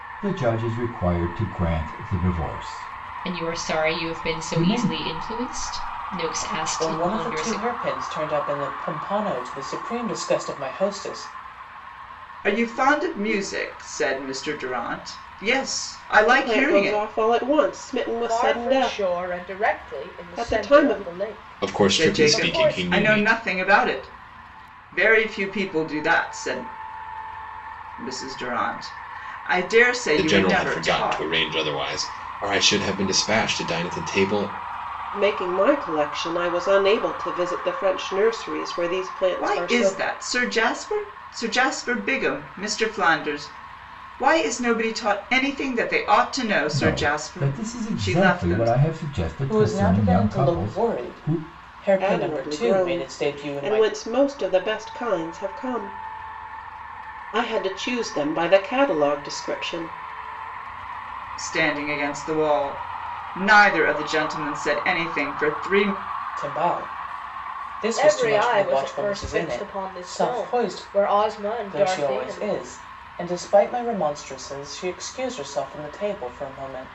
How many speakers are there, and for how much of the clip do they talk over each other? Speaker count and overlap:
7, about 26%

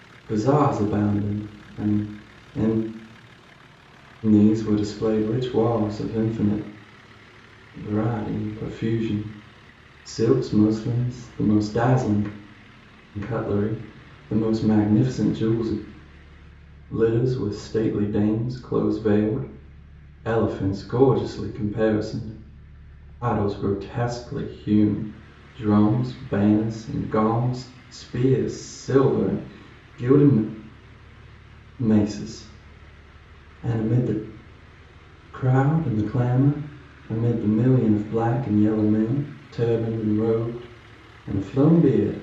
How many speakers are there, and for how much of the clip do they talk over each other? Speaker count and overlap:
1, no overlap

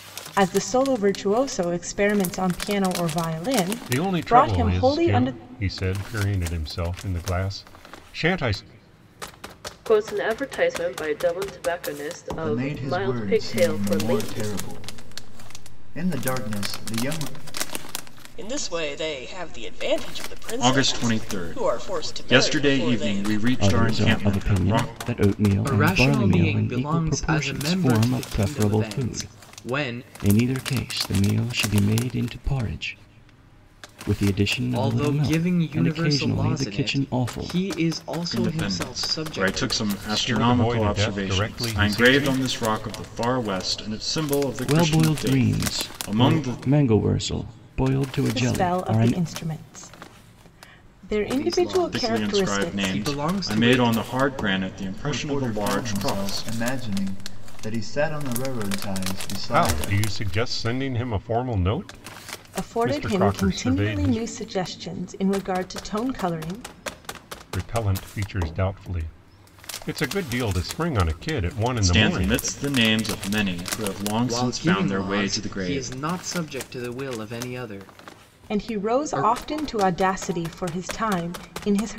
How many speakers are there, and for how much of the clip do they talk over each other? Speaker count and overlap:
8, about 39%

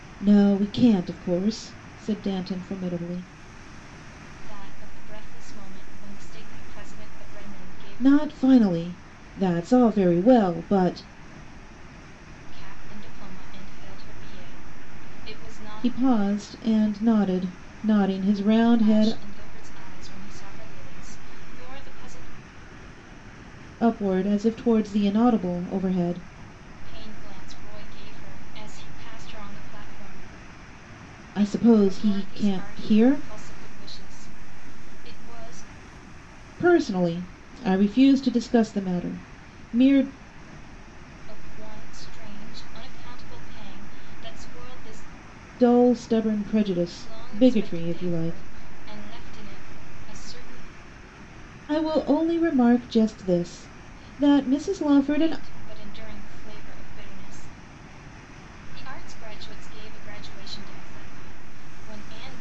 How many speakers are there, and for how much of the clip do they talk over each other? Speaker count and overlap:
2, about 7%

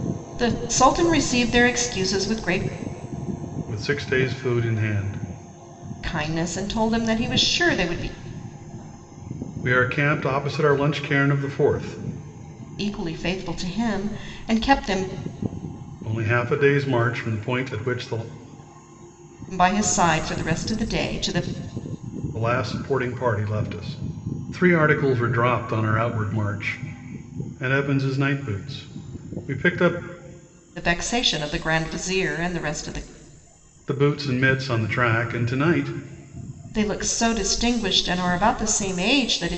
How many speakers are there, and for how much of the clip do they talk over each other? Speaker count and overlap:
2, no overlap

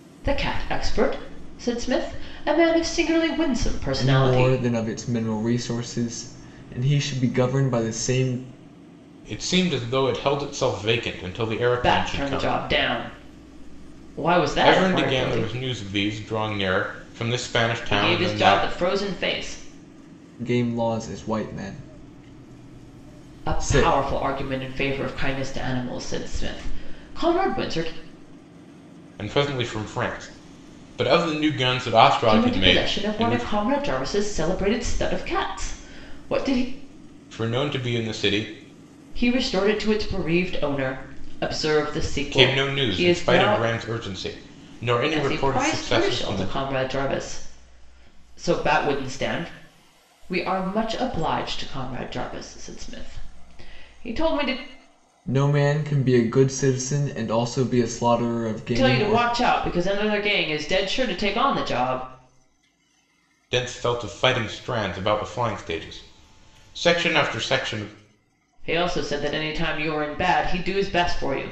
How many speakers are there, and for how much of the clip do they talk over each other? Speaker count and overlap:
3, about 12%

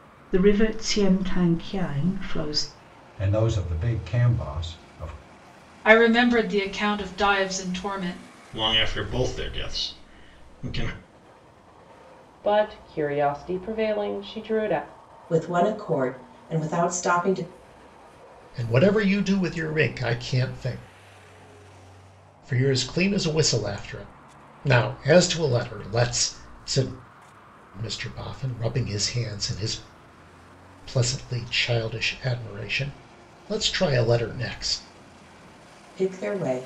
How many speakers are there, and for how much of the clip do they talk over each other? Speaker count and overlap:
7, no overlap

